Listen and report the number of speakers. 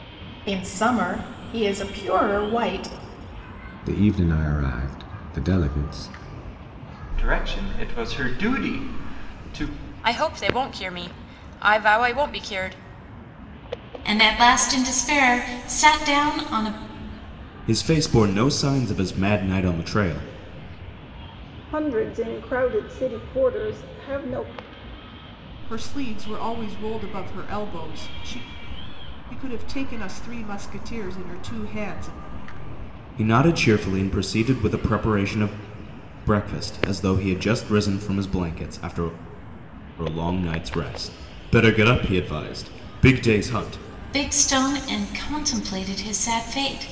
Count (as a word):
eight